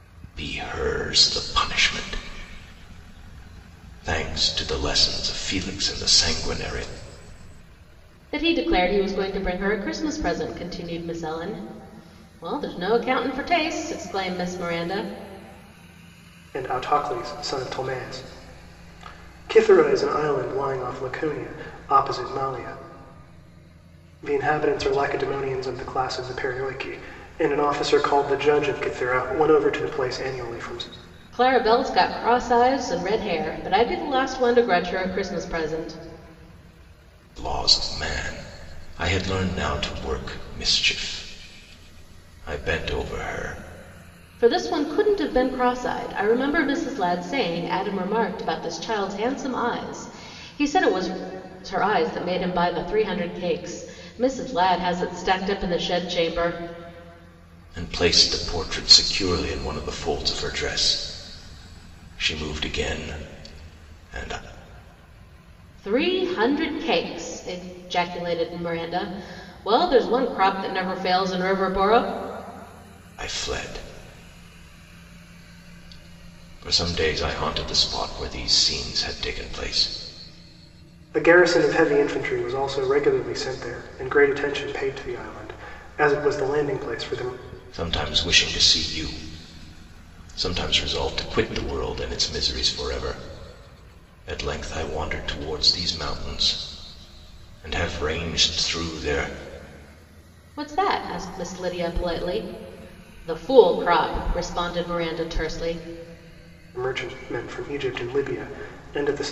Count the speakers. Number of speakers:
3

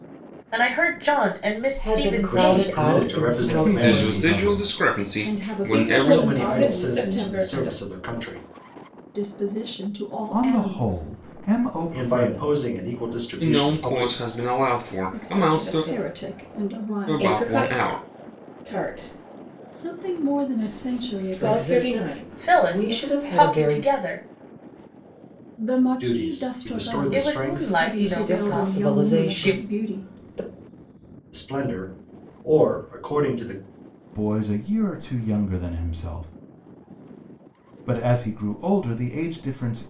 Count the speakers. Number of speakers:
7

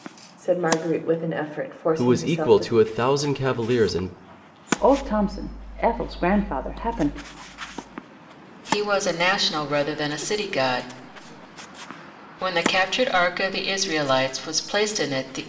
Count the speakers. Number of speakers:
4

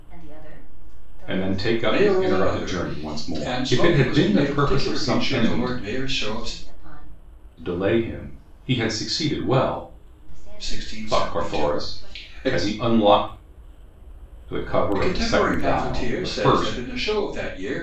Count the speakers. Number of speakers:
3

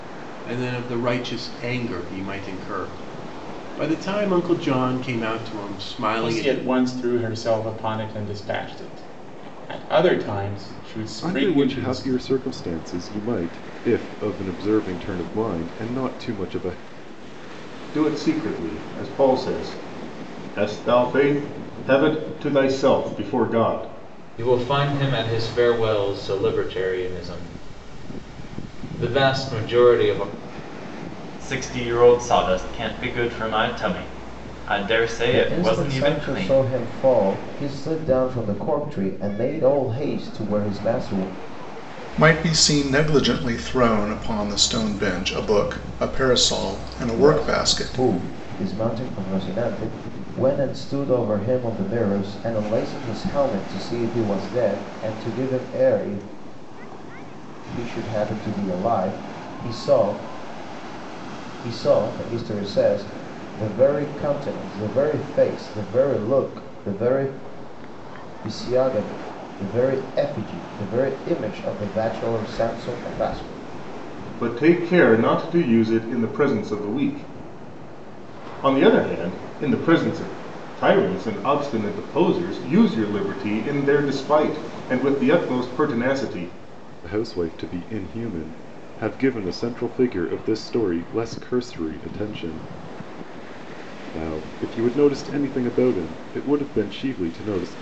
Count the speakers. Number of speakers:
8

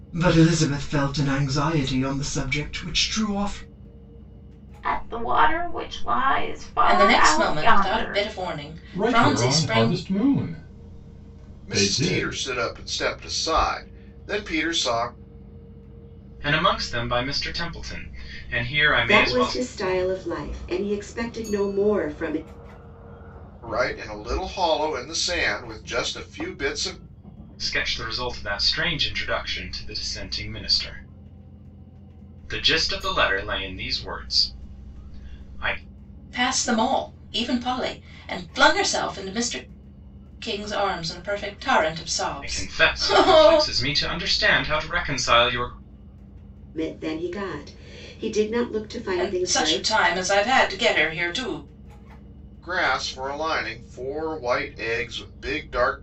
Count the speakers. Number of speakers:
7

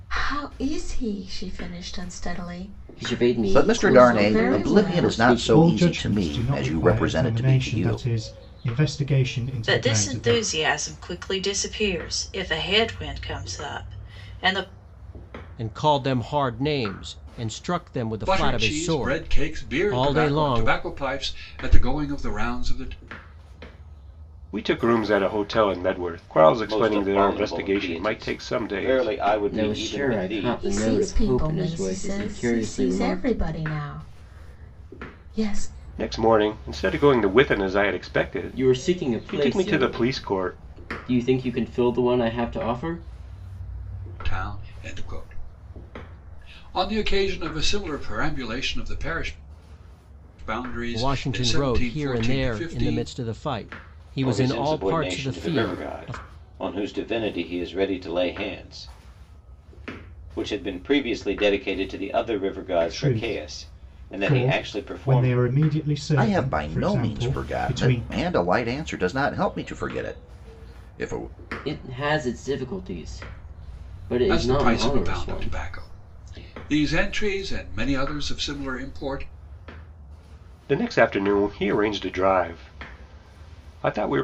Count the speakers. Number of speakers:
9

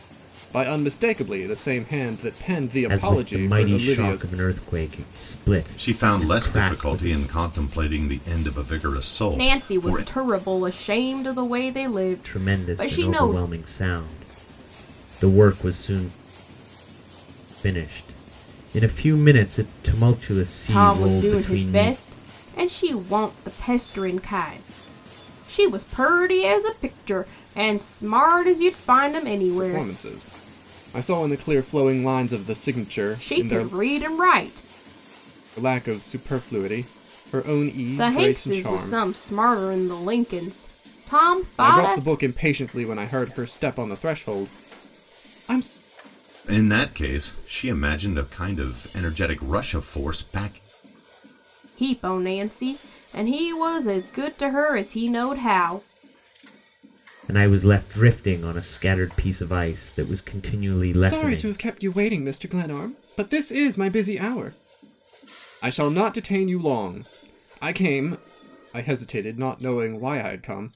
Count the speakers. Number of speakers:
4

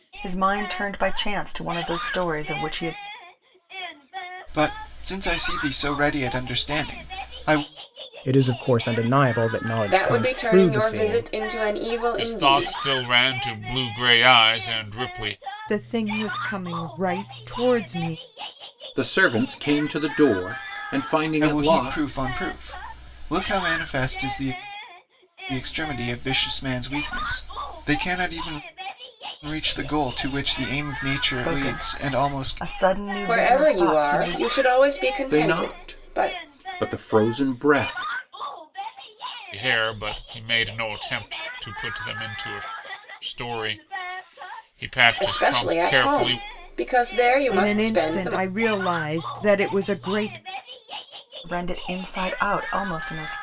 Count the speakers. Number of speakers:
7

